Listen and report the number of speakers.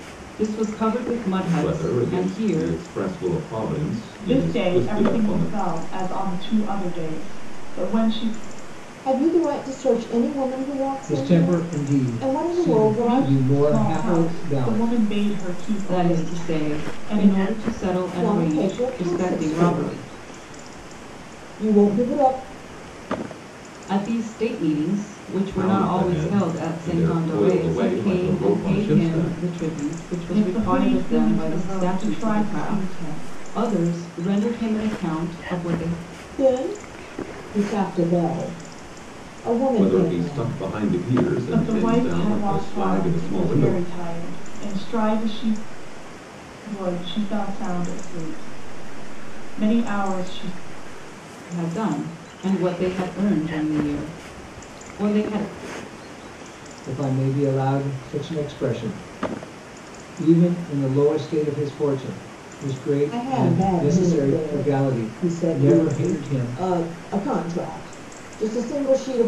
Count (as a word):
five